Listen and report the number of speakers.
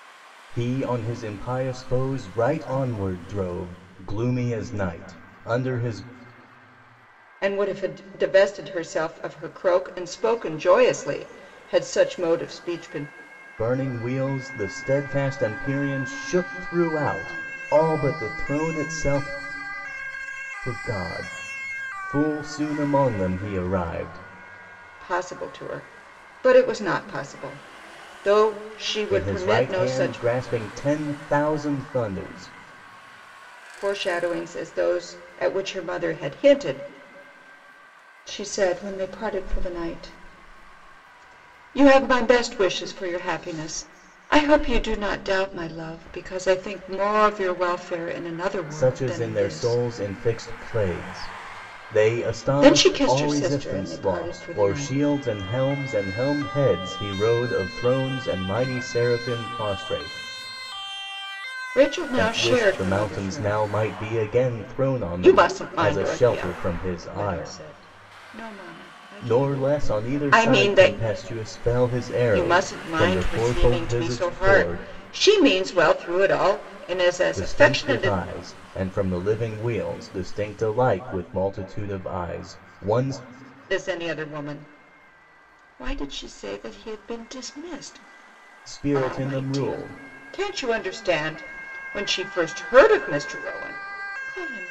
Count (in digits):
2